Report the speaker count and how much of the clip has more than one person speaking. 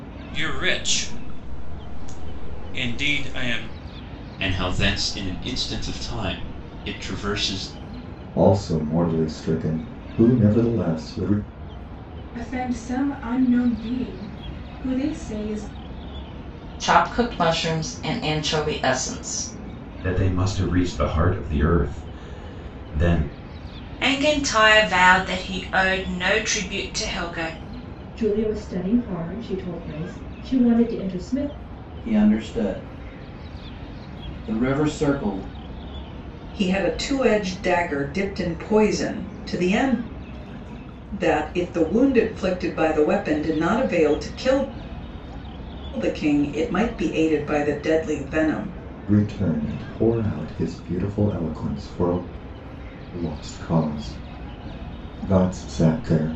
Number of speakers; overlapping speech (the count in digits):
10, no overlap